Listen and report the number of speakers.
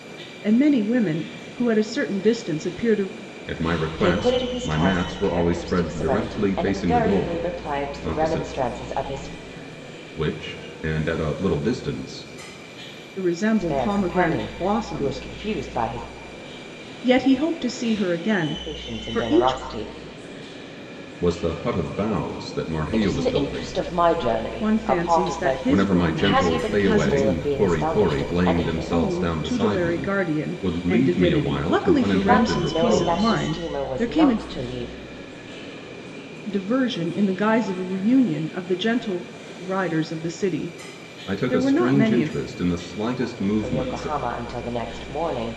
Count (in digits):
3